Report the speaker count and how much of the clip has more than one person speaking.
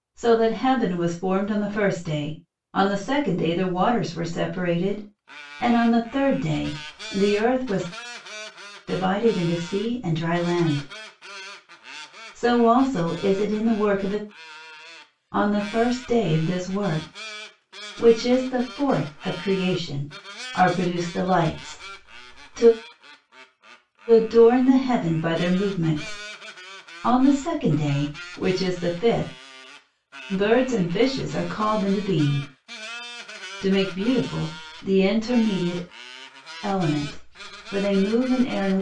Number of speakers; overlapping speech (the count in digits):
1, no overlap